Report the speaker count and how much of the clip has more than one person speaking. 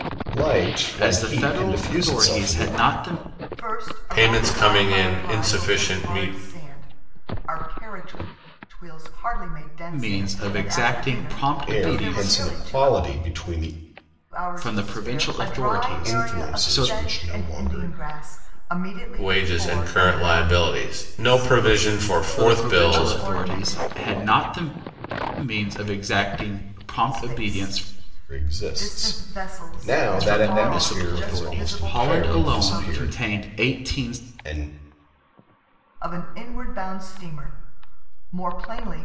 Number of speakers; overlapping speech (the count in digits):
4, about 56%